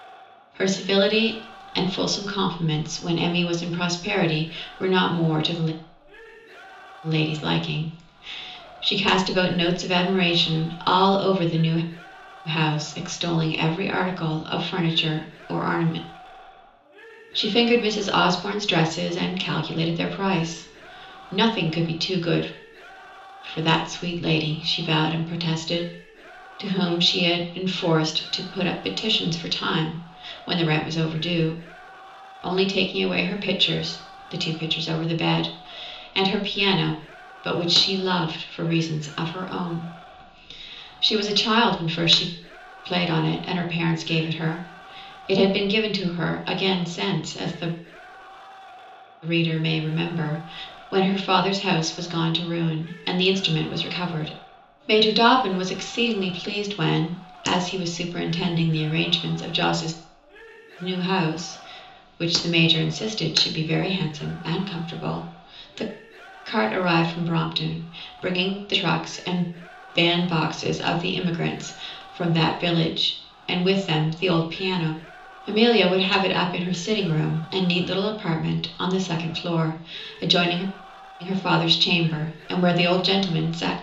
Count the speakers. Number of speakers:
one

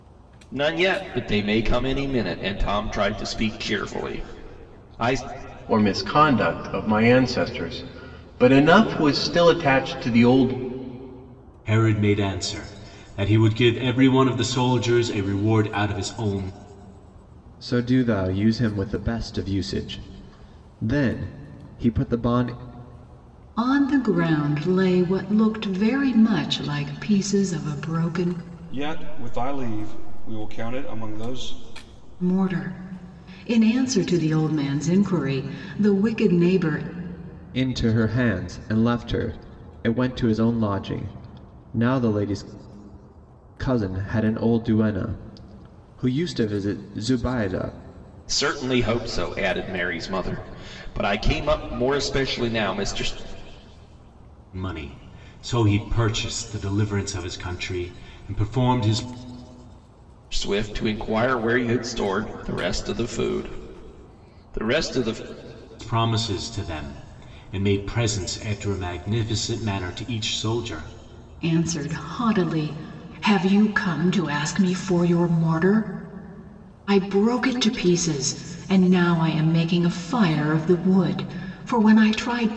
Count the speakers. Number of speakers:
six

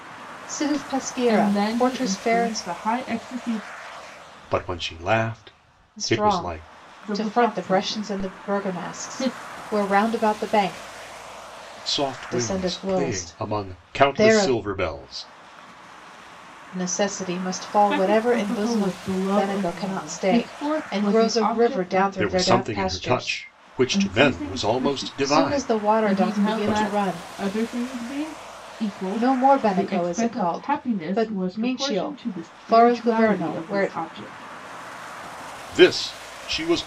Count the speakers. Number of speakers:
three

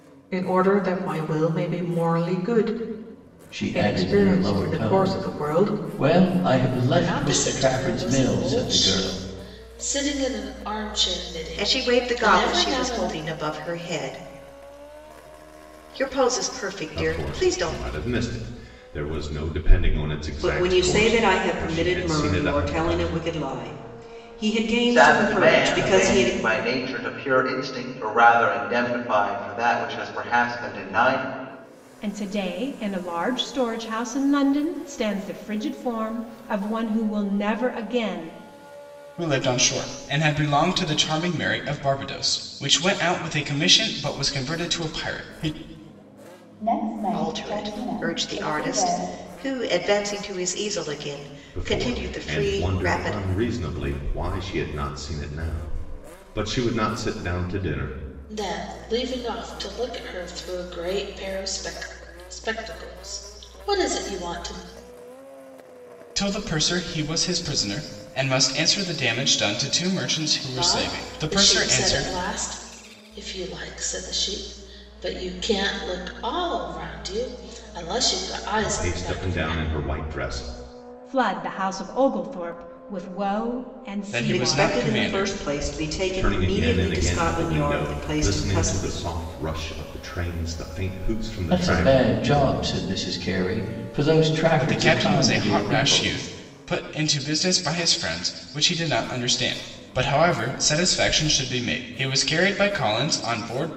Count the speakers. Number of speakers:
ten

